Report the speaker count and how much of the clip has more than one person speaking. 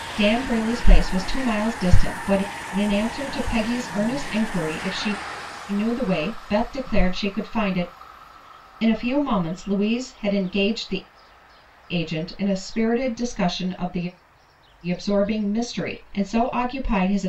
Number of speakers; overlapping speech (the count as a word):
one, no overlap